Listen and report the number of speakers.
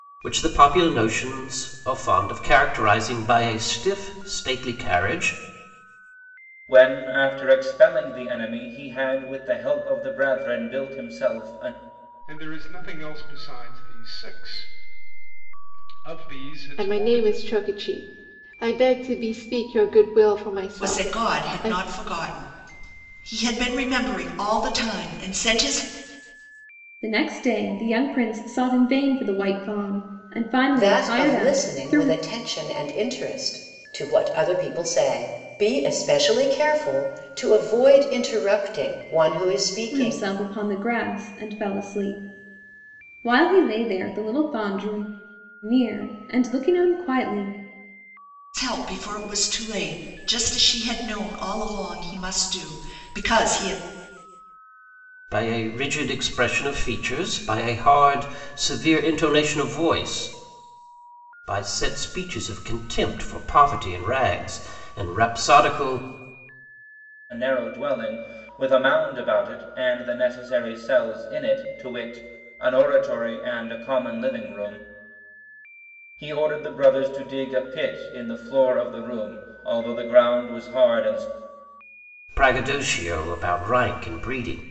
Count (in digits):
7